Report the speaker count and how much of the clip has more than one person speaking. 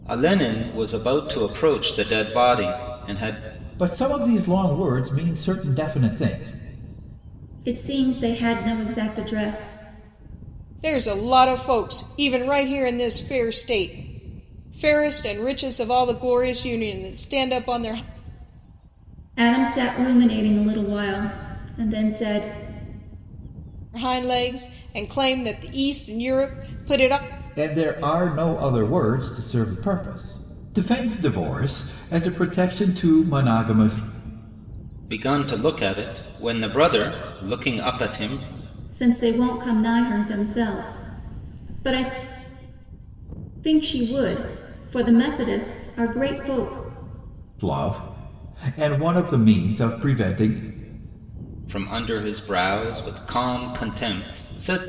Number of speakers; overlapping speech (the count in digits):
4, no overlap